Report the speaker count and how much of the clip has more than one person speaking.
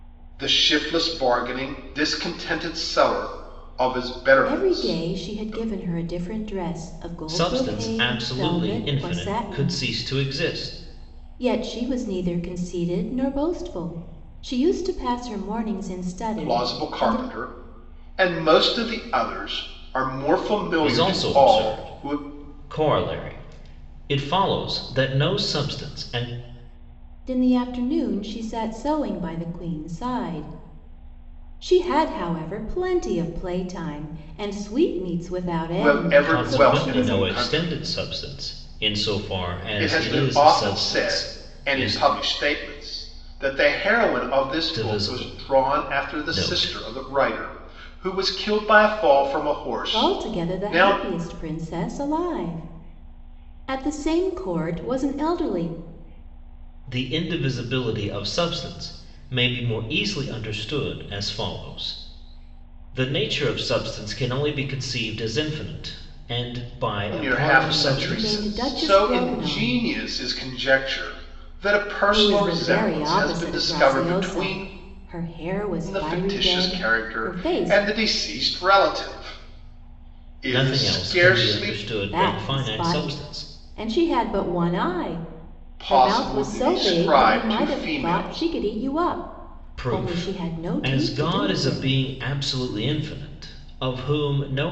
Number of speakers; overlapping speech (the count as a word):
three, about 30%